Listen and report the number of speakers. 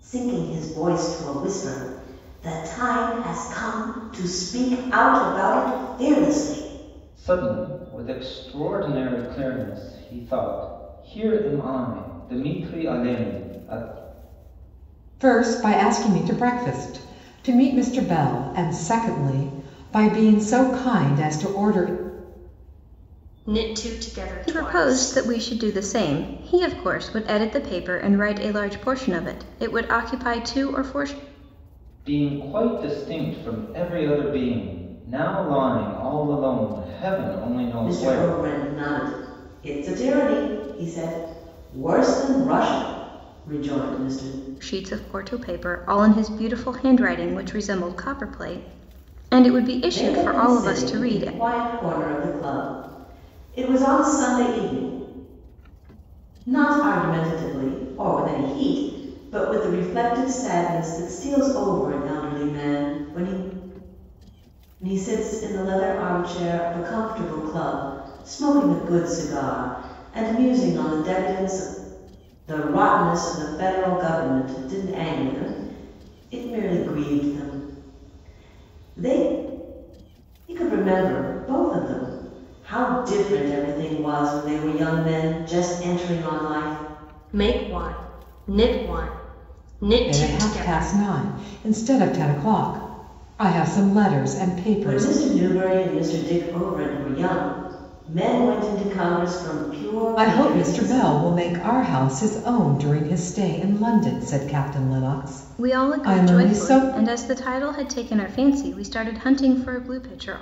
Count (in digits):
5